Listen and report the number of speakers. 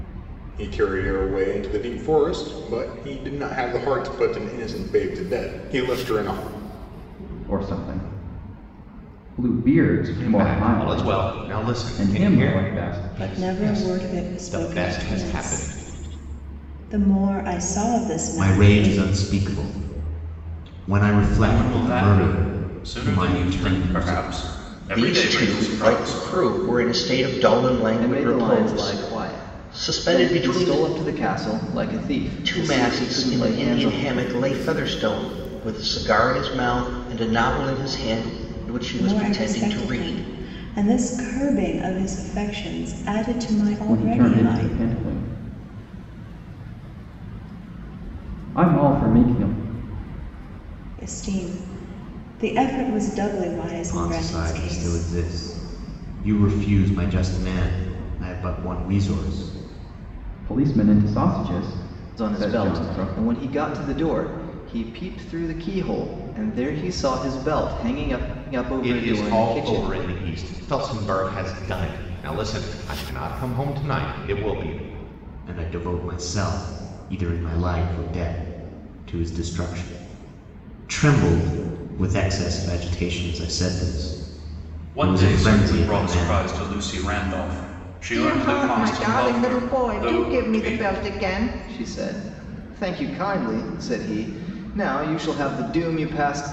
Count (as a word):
eight